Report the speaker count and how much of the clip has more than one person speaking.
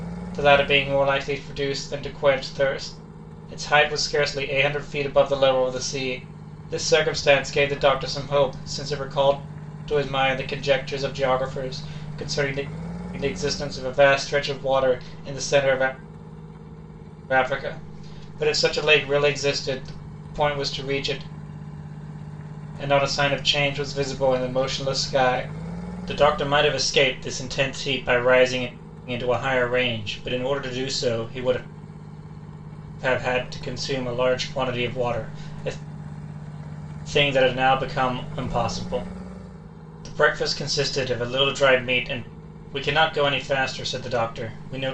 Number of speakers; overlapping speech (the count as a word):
one, no overlap